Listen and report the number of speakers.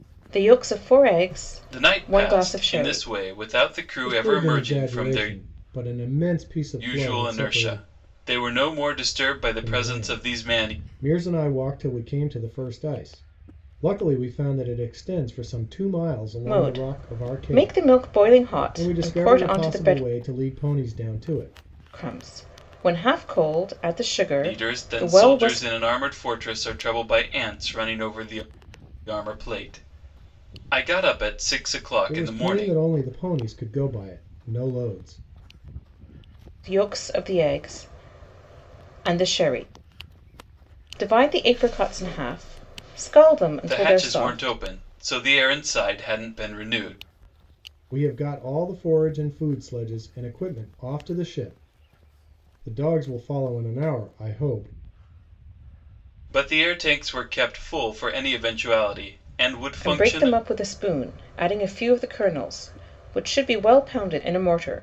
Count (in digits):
3